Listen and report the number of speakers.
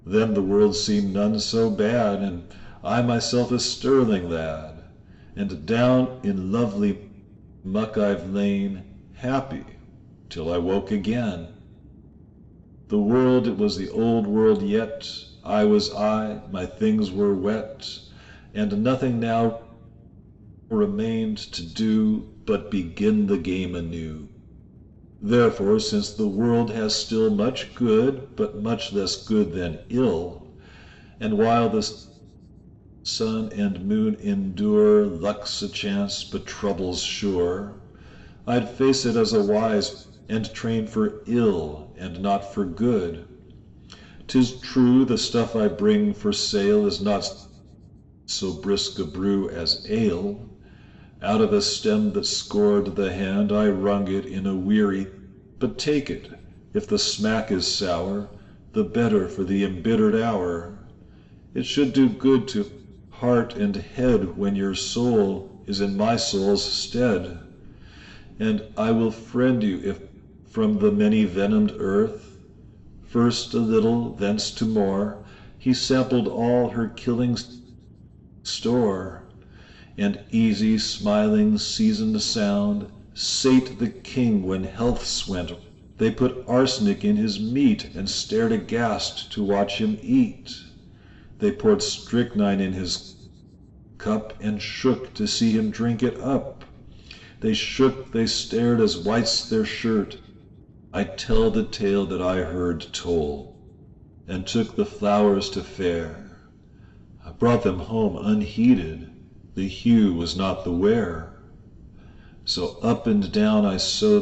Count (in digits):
1